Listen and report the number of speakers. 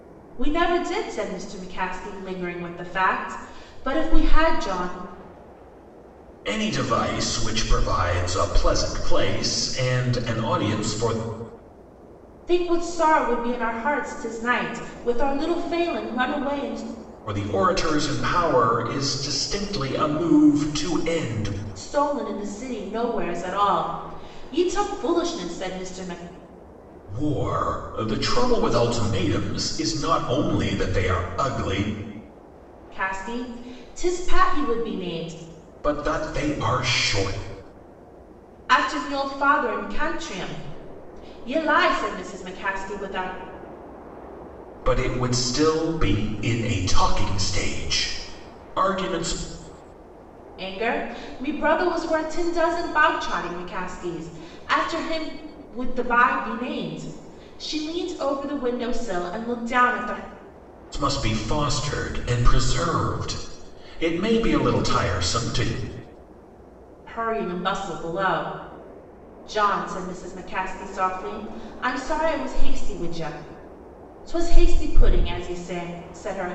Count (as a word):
two